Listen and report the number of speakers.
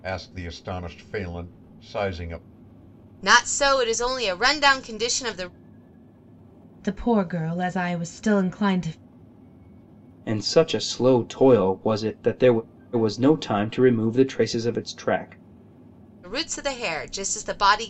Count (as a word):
four